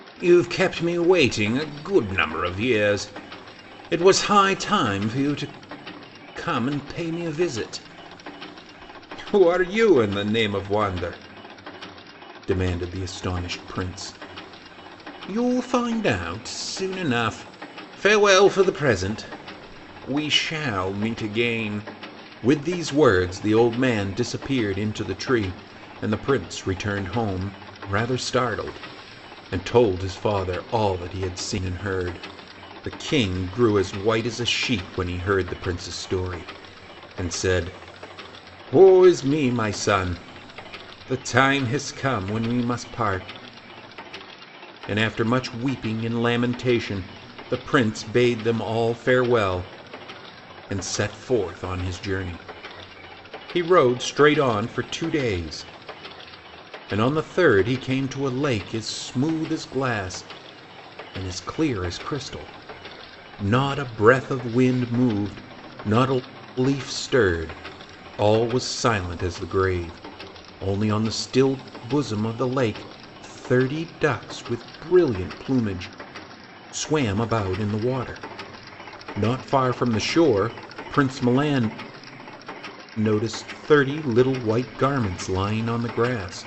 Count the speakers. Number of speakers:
1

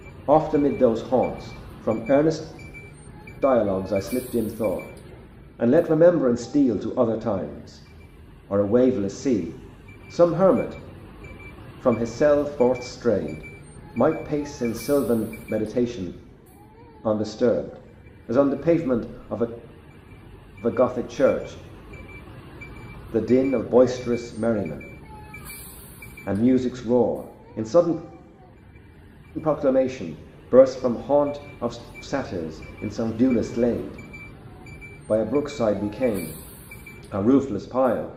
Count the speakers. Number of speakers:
1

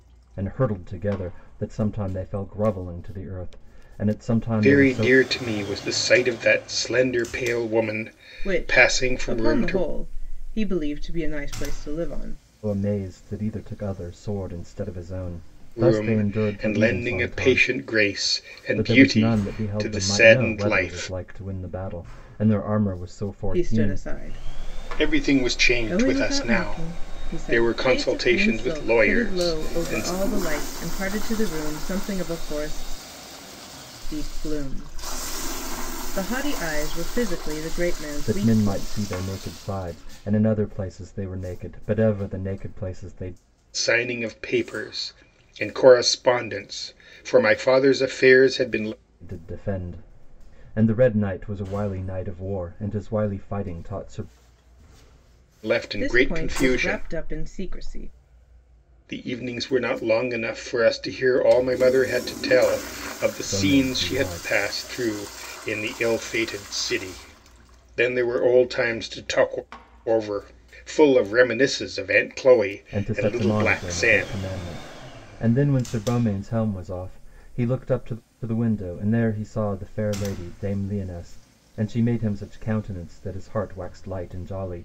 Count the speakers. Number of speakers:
3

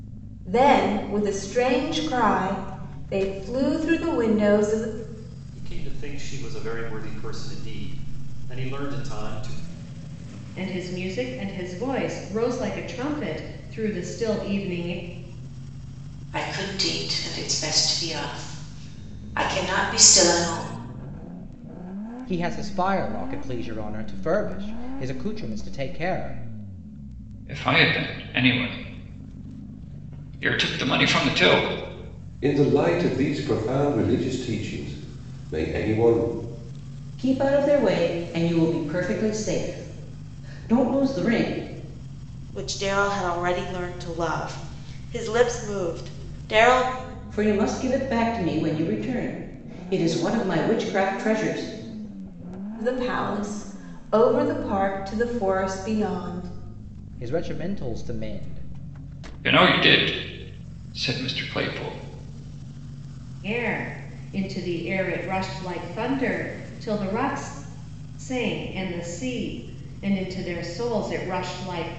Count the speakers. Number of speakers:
9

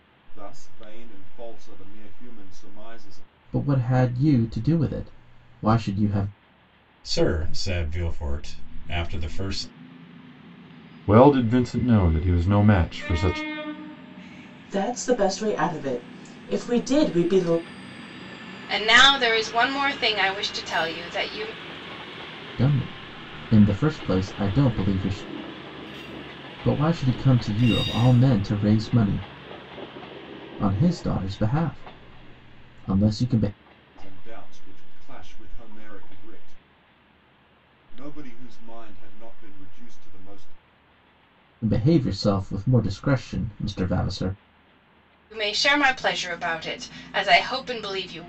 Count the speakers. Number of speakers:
6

